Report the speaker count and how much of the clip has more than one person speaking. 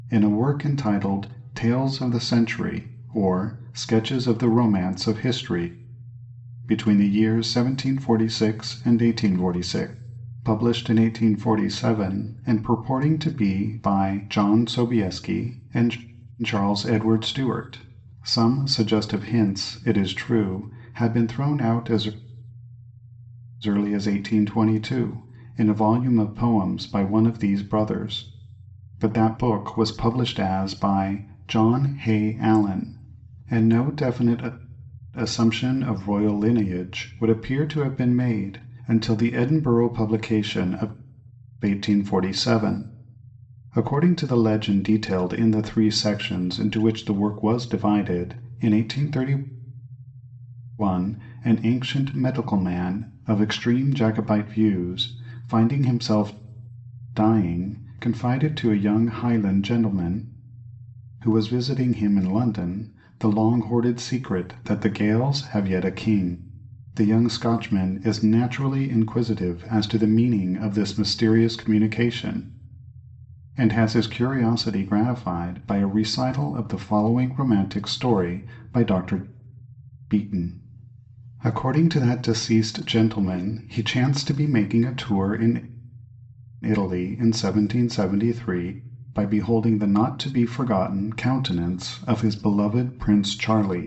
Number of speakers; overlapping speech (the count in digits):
1, no overlap